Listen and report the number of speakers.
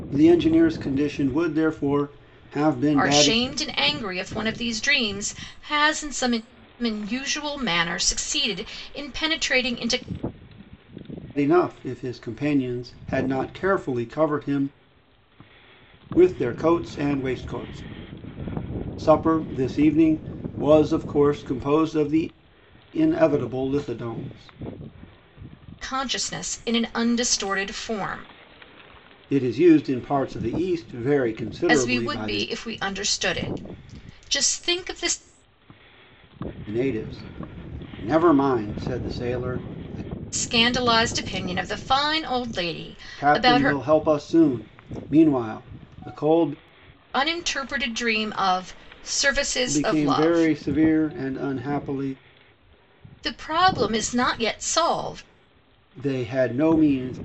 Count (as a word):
two